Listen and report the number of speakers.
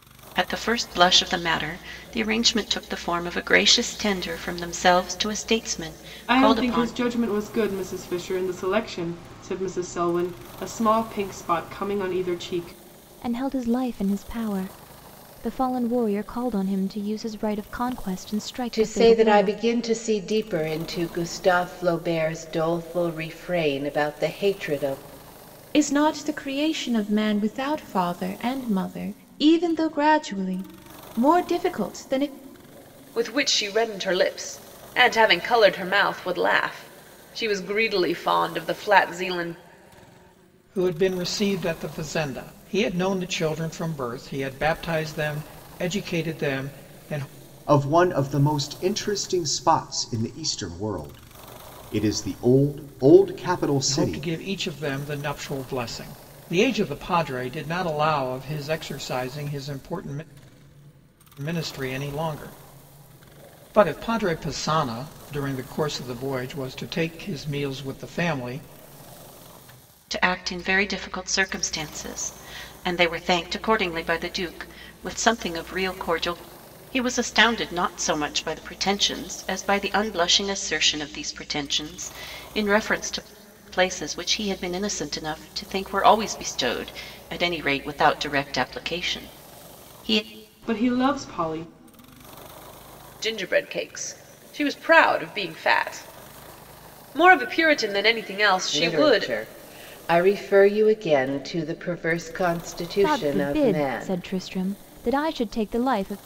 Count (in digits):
8